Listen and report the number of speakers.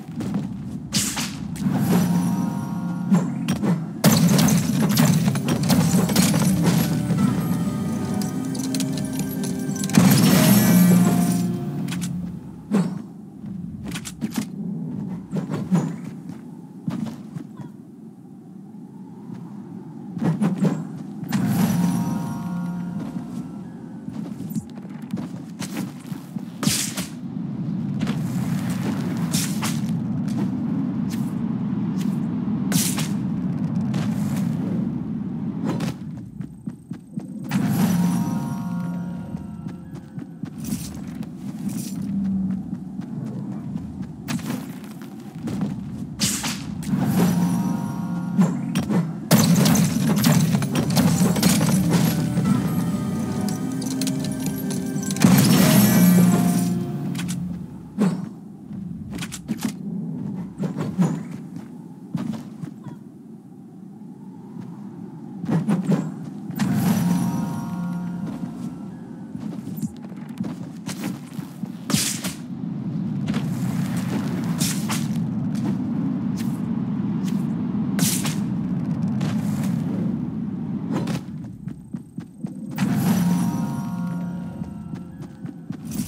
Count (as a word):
zero